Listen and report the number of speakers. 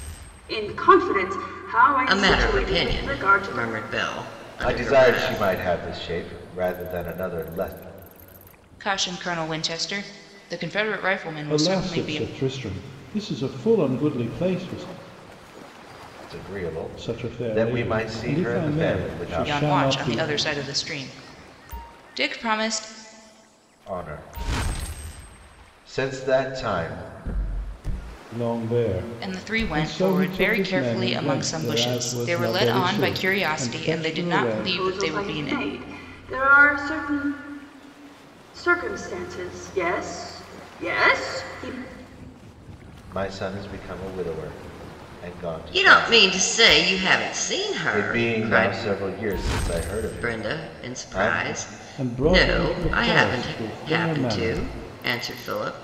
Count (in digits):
5